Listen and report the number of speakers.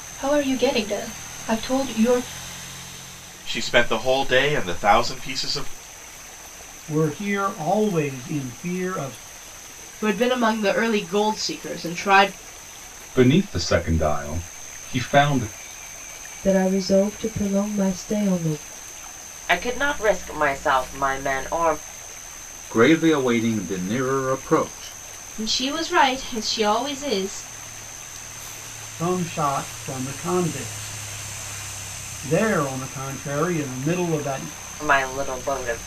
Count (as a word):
nine